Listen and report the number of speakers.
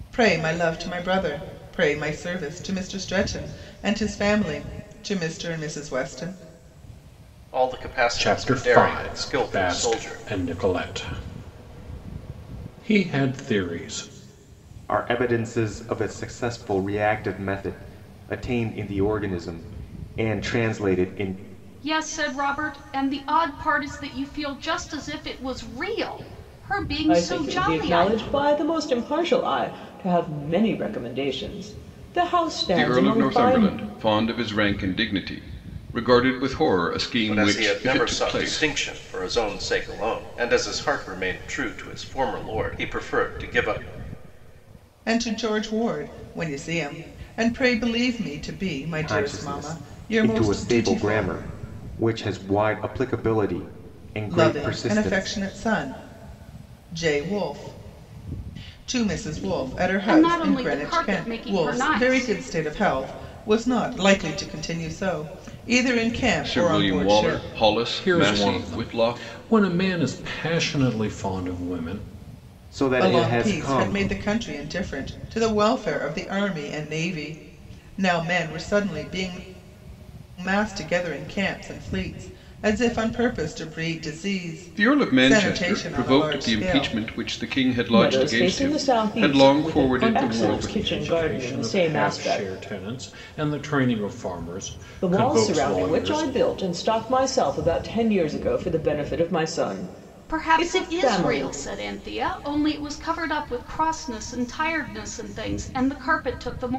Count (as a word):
seven